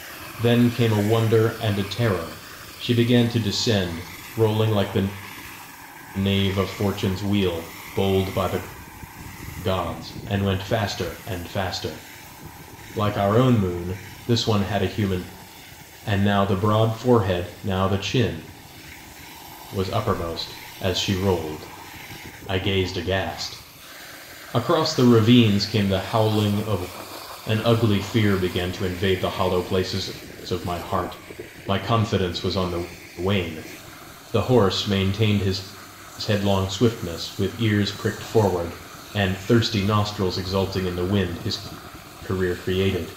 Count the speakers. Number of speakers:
one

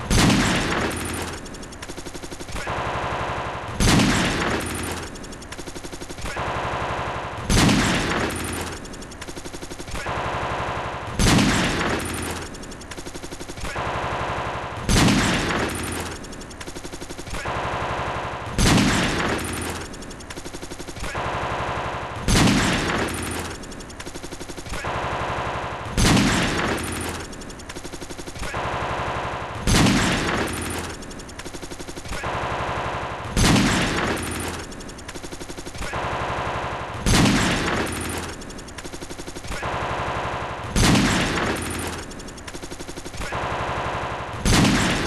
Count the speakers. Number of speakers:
zero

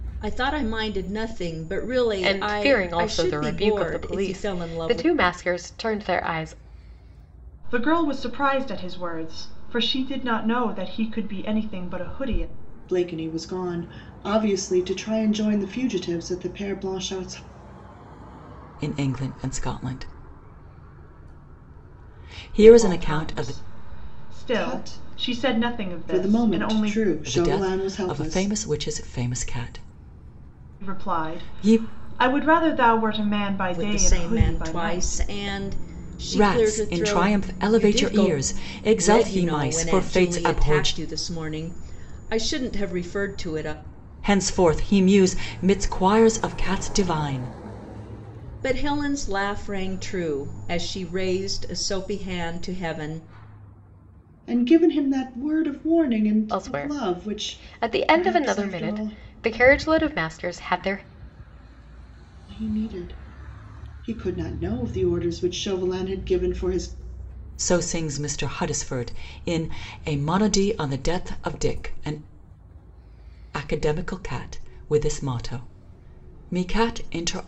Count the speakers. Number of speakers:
five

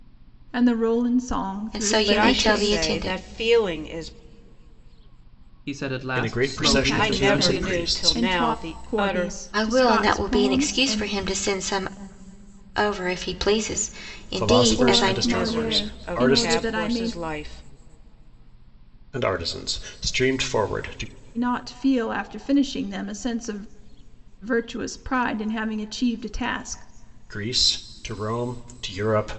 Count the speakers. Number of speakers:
five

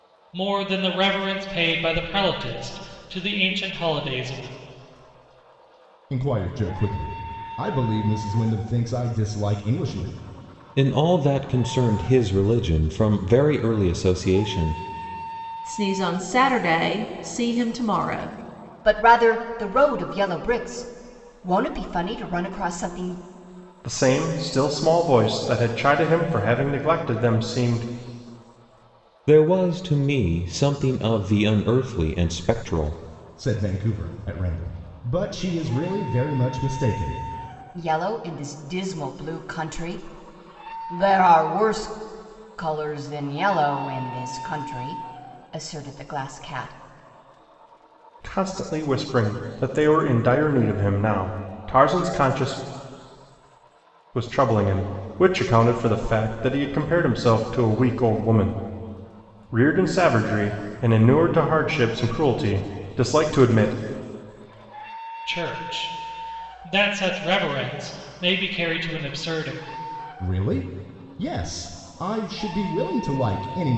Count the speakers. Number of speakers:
six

